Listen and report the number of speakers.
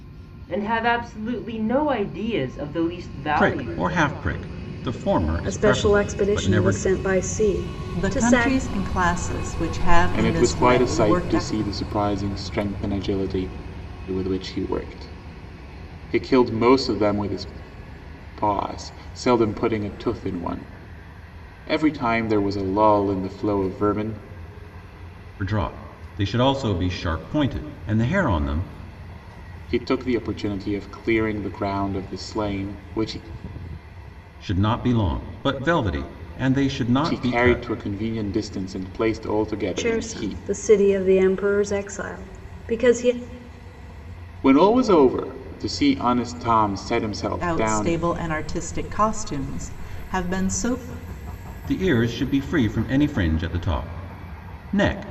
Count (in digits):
5